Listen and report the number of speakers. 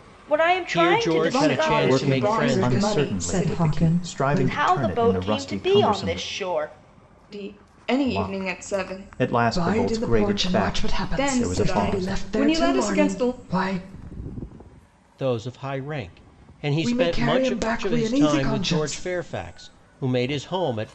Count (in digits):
5